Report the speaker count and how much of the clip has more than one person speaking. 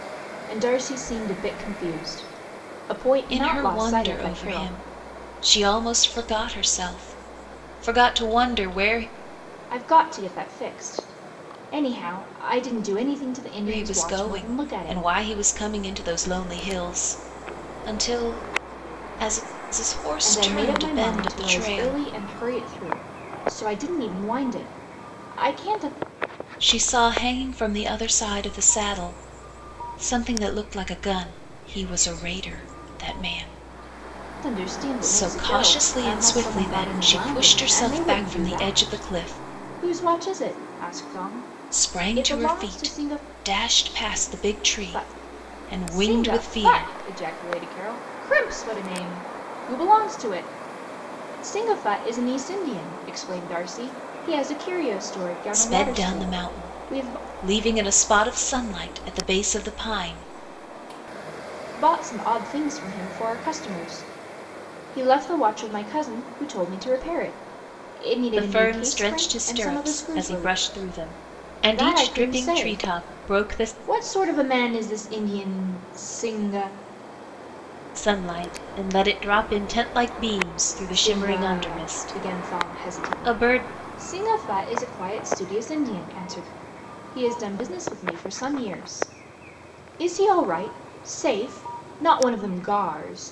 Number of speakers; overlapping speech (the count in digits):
2, about 24%